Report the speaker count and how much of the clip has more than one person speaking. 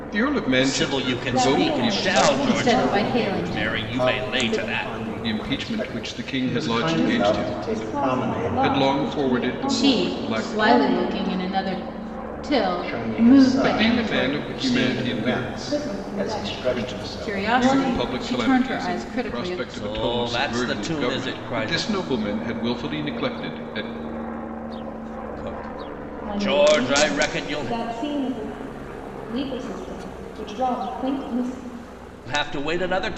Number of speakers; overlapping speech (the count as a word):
five, about 64%